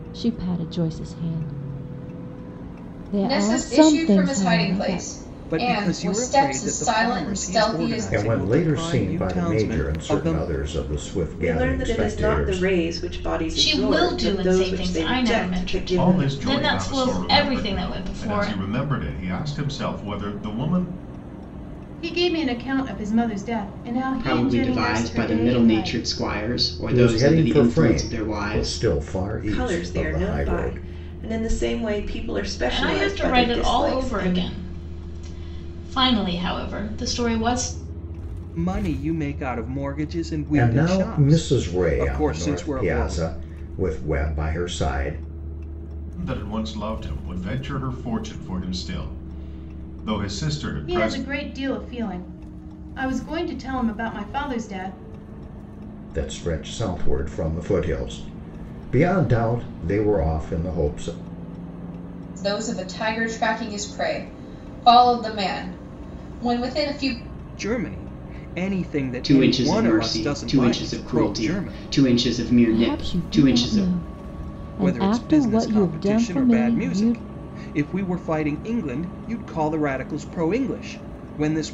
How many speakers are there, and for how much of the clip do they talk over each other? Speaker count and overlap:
nine, about 37%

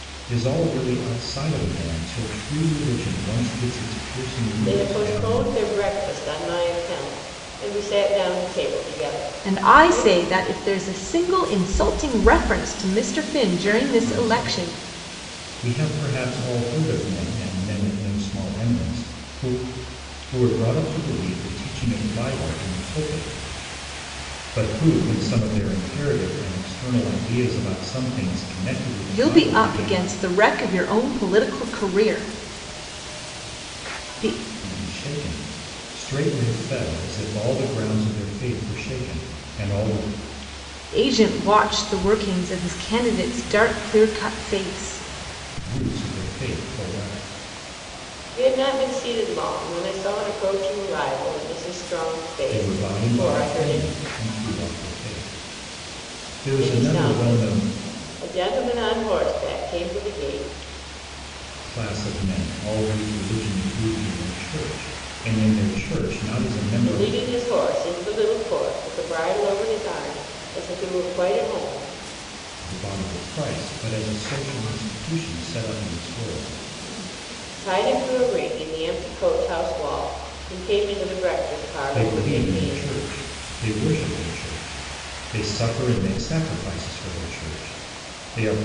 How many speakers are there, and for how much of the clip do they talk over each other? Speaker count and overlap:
three, about 8%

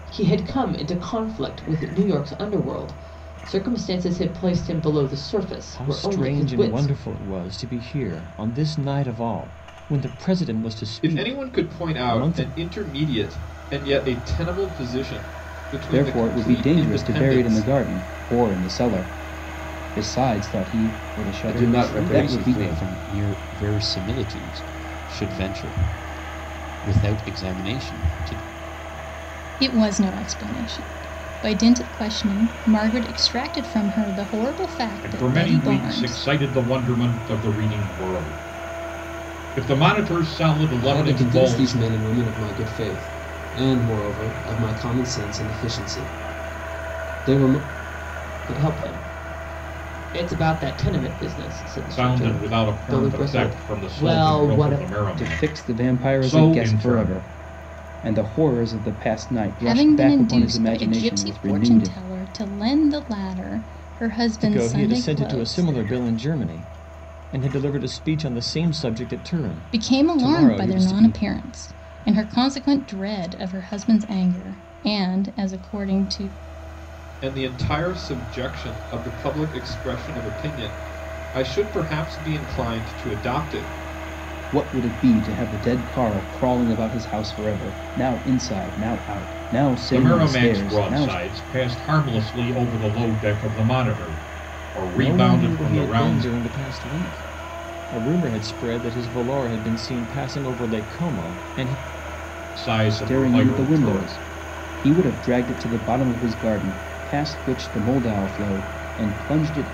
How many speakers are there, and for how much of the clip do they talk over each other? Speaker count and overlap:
nine, about 21%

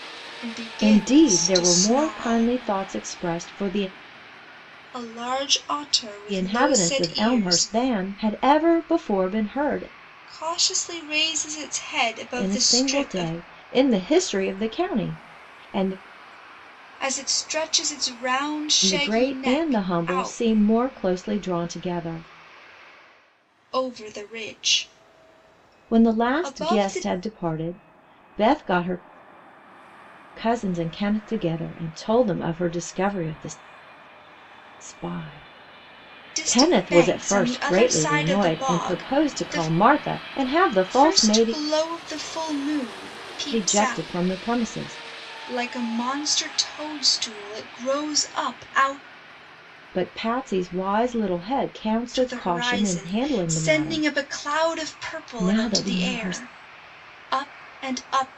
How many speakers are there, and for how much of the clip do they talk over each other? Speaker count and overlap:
two, about 28%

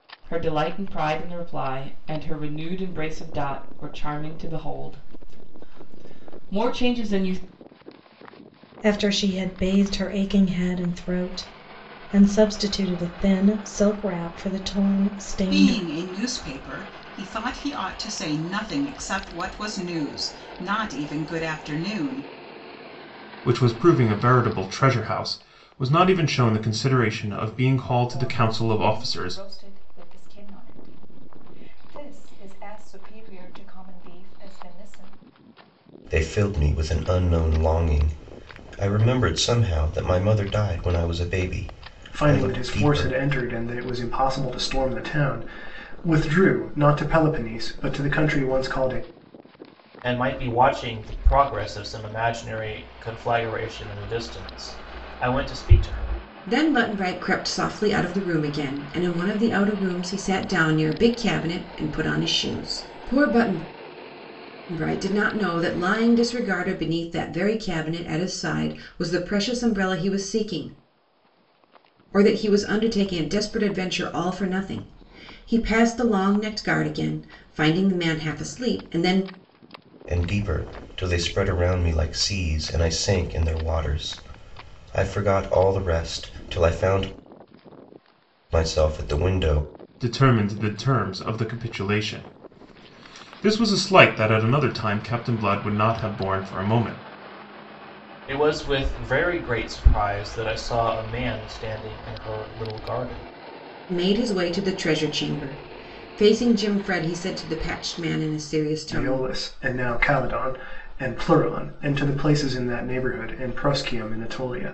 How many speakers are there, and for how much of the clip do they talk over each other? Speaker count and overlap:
nine, about 3%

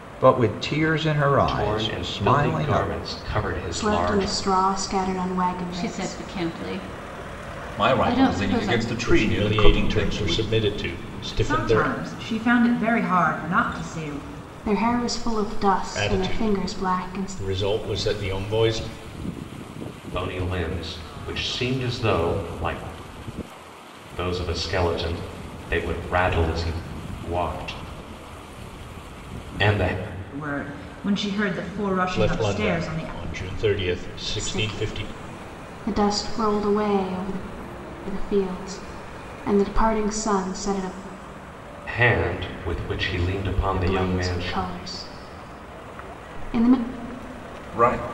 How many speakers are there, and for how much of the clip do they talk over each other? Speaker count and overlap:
seven, about 20%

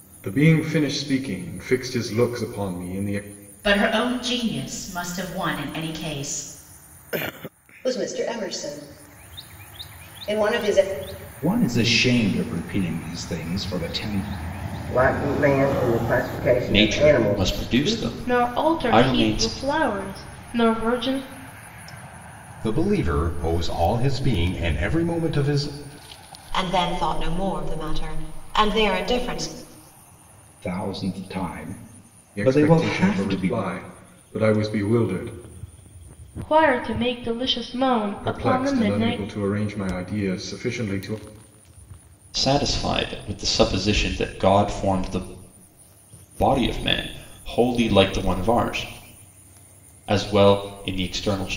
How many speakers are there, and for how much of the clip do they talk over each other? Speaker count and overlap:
nine, about 10%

